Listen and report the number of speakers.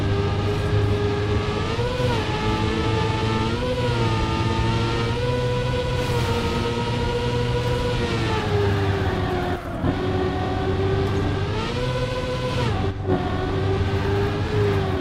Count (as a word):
zero